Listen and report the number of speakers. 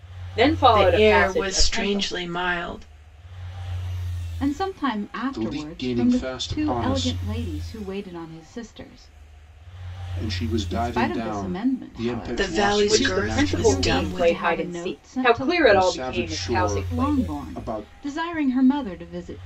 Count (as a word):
four